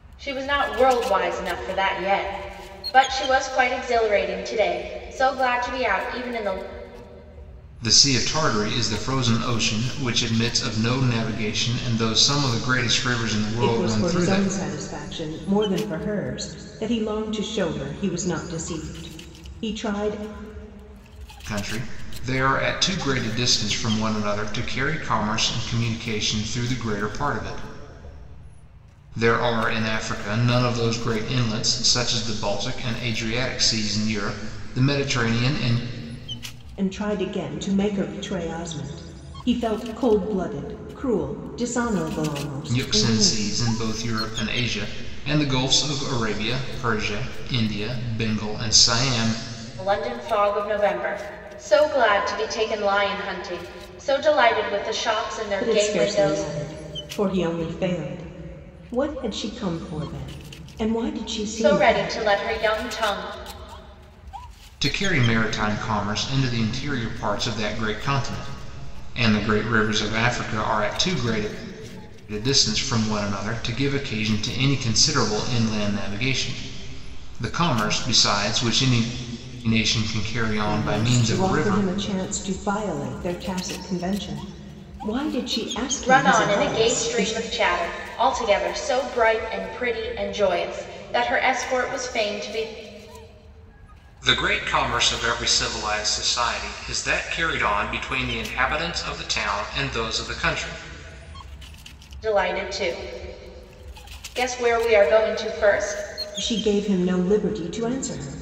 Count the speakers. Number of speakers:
3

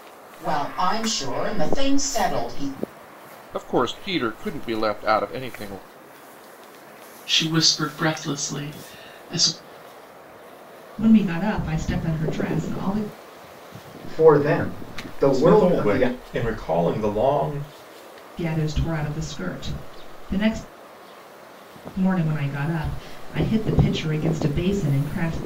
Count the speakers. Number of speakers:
6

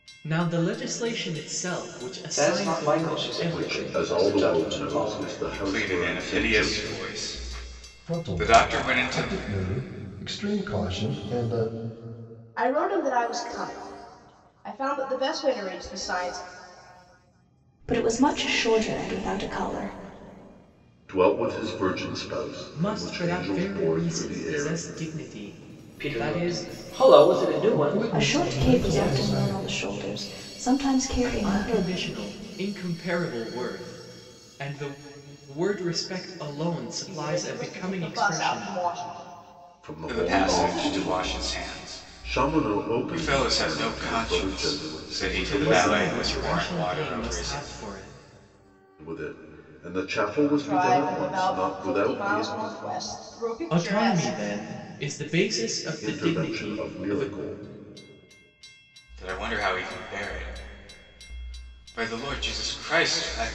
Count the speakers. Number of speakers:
7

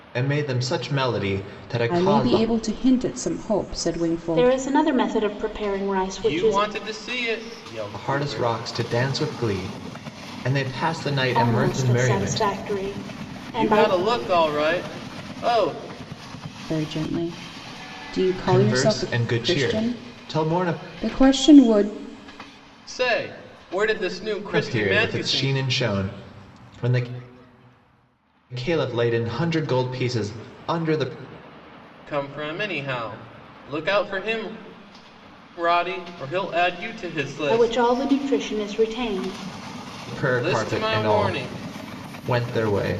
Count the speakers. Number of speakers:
4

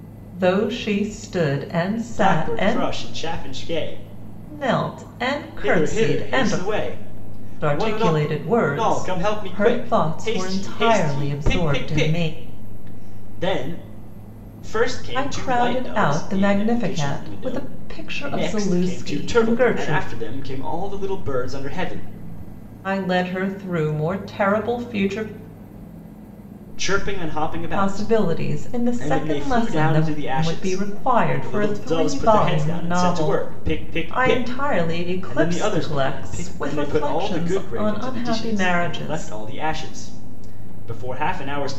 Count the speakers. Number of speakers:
2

